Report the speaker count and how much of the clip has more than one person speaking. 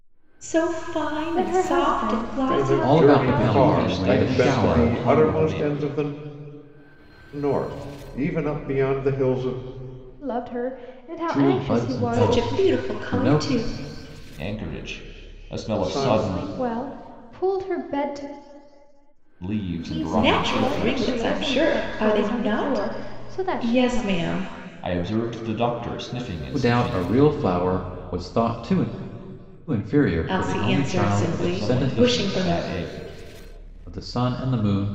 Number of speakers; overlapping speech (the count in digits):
5, about 42%